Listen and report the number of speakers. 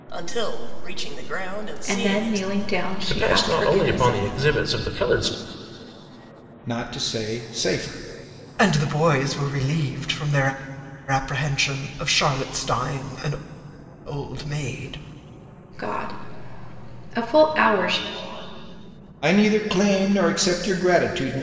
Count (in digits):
5